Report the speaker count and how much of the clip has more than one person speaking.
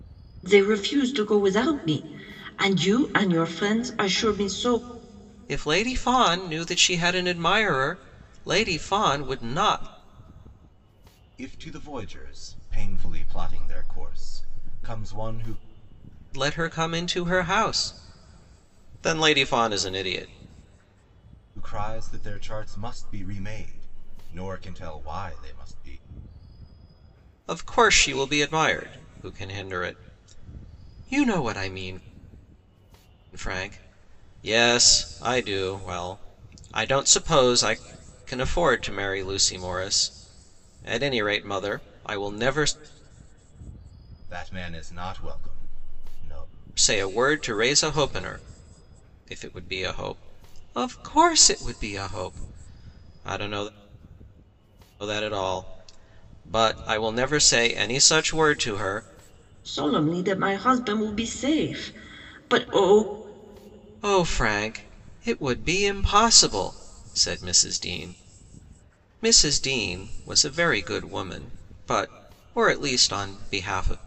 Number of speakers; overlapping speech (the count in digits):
3, no overlap